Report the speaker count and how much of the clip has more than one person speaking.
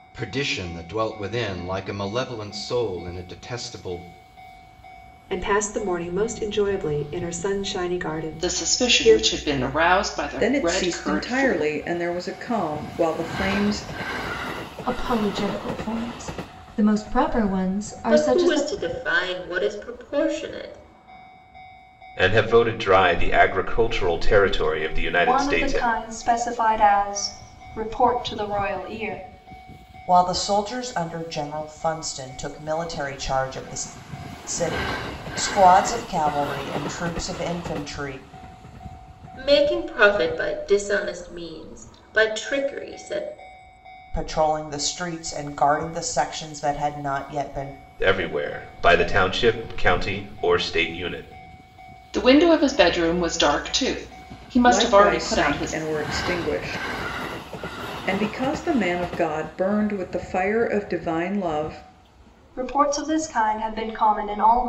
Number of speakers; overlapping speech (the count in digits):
9, about 7%